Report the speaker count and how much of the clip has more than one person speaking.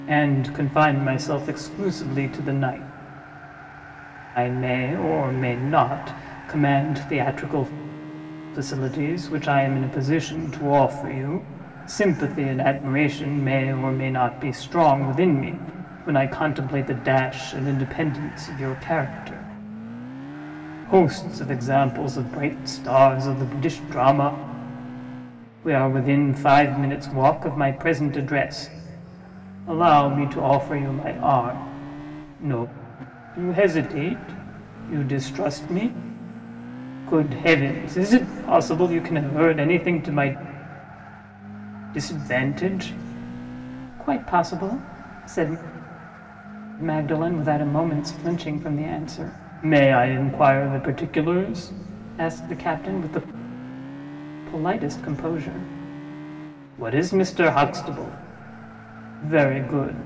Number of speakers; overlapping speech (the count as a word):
one, no overlap